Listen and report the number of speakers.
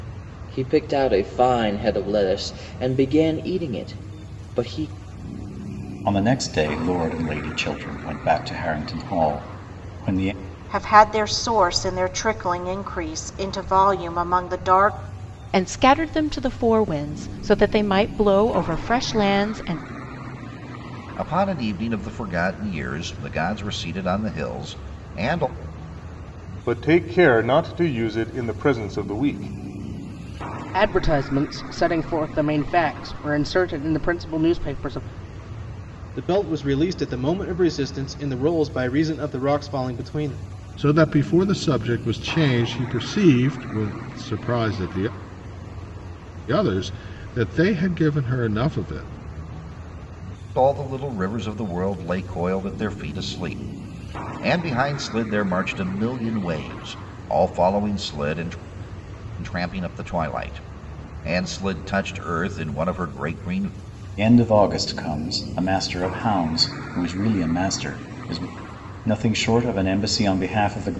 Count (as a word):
nine